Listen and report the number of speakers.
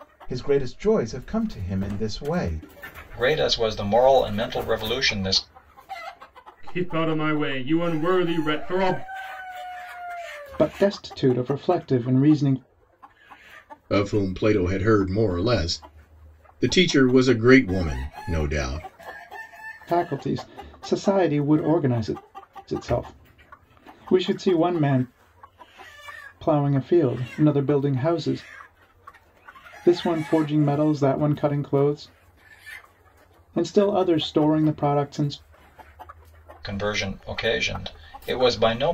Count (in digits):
5